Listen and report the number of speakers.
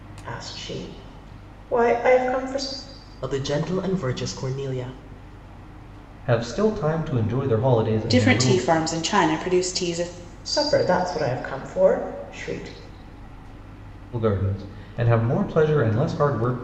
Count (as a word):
four